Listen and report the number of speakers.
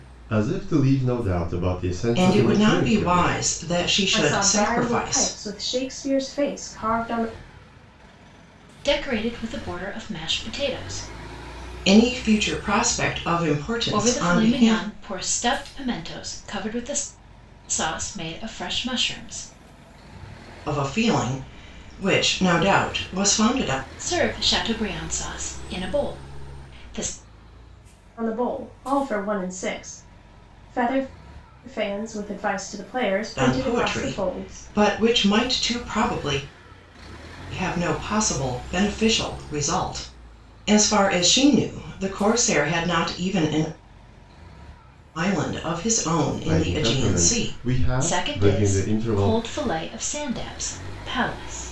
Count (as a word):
four